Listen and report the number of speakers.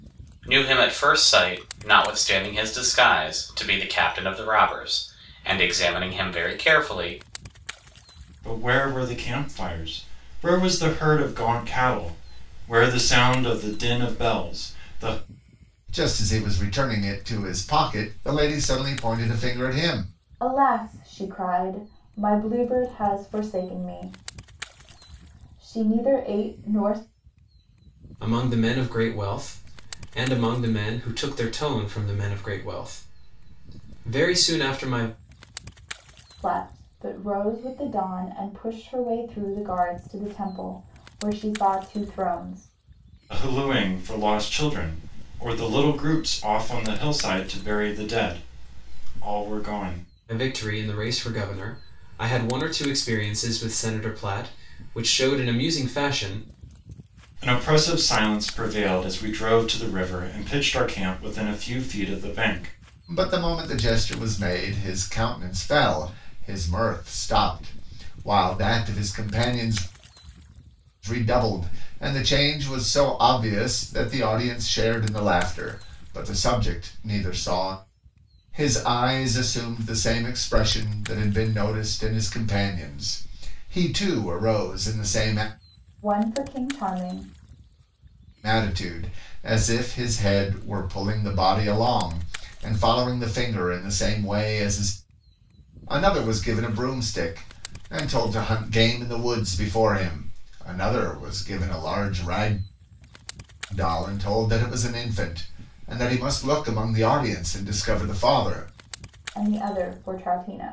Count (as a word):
five